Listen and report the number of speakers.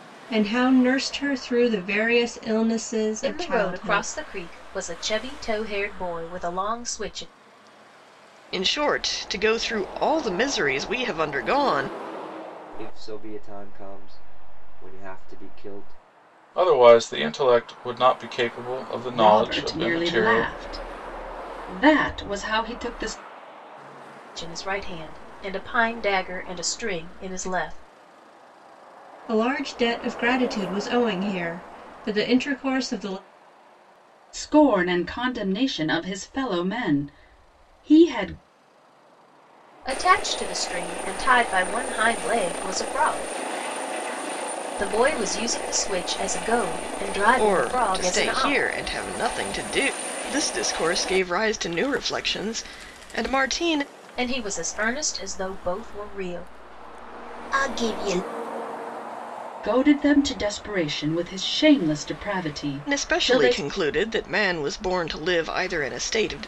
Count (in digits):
6